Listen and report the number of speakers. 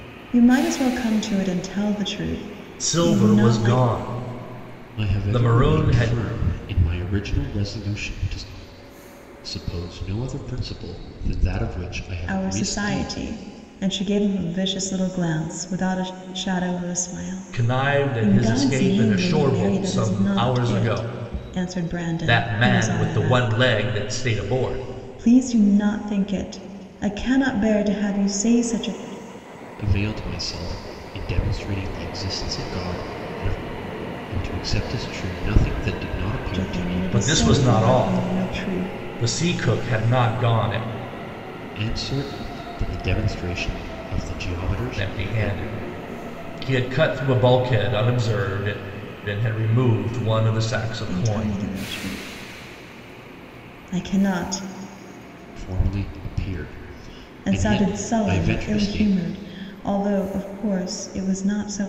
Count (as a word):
three